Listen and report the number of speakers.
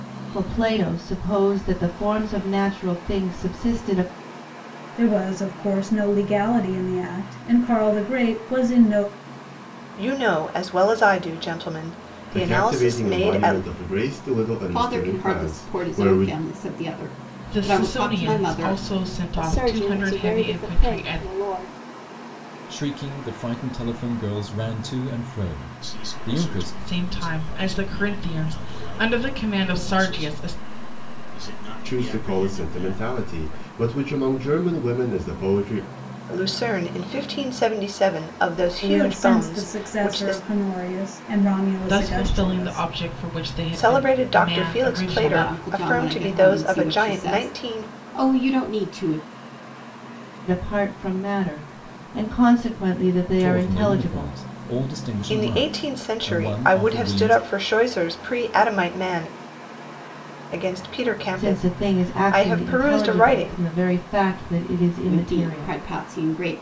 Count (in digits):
9